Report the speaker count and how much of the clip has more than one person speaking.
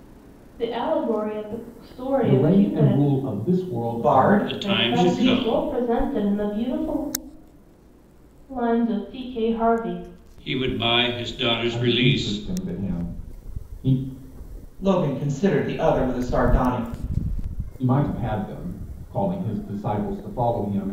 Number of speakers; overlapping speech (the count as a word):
four, about 15%